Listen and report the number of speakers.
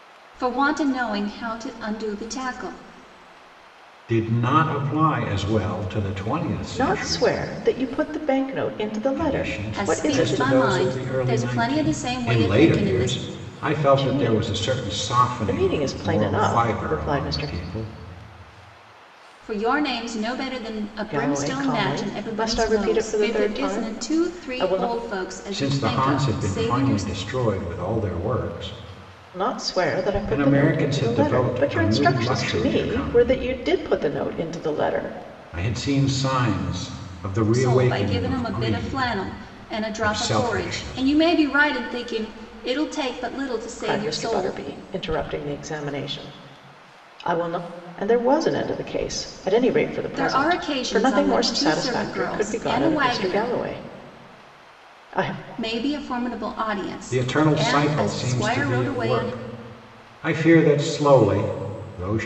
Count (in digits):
3